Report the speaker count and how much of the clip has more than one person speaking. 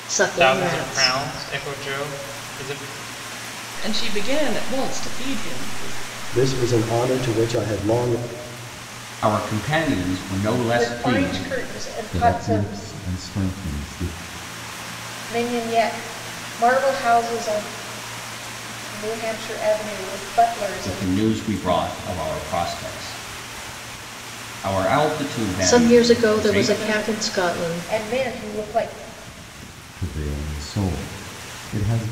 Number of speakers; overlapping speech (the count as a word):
seven, about 16%